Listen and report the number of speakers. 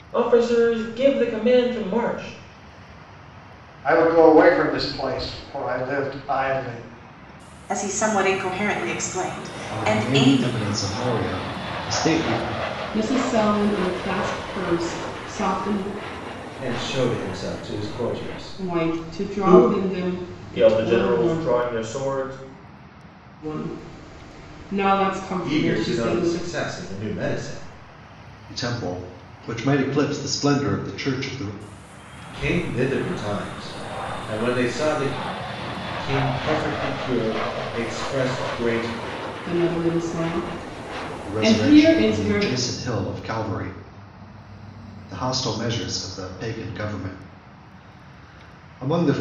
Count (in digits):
6